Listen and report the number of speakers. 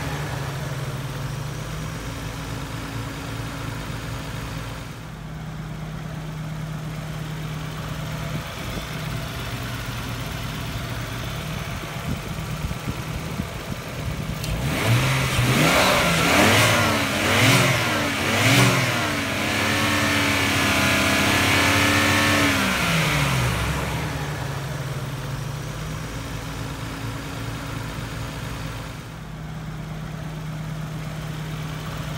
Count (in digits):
0